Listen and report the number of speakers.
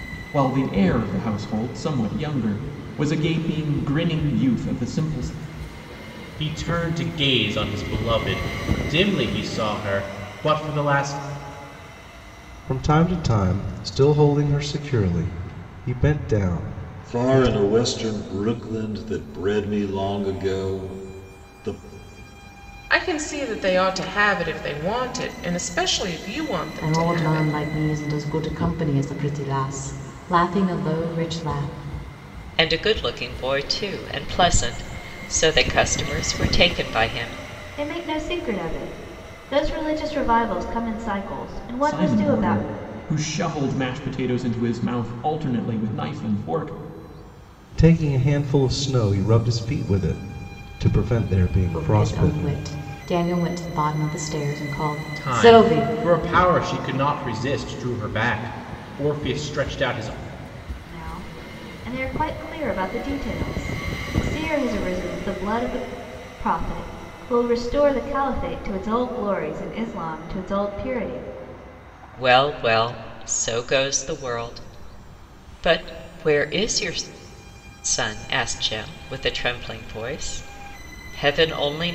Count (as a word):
eight